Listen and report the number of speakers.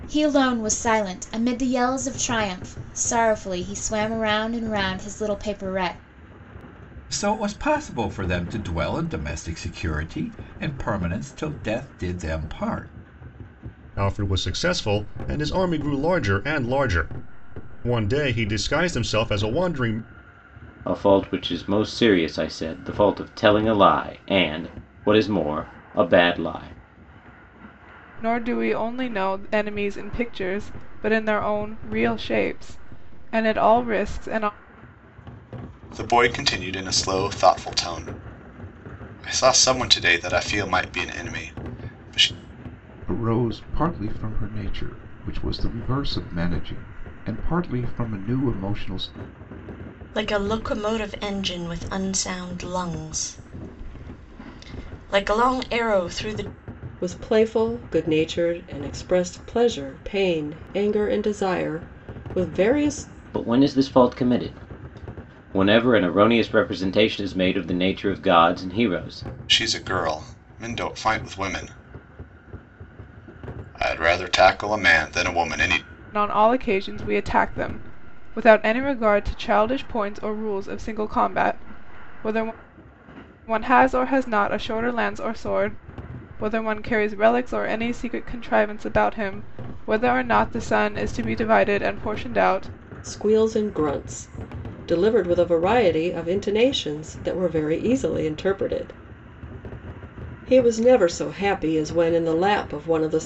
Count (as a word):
nine